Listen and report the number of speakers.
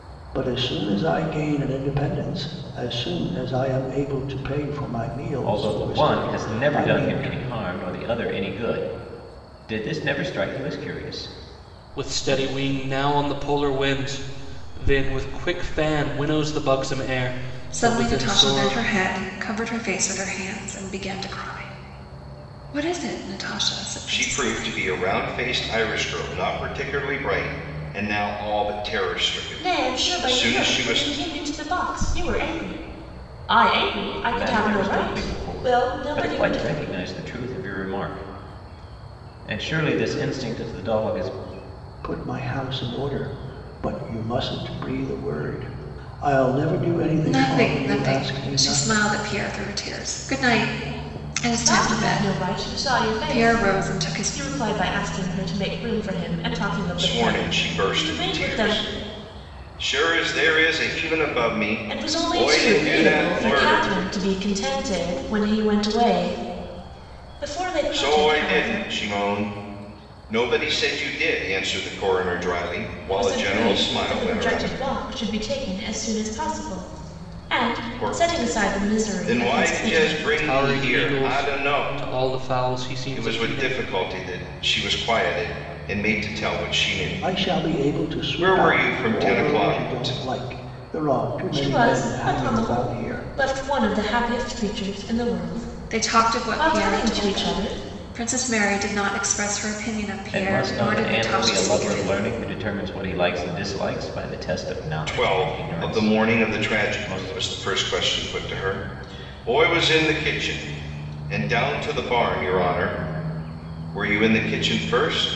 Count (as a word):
six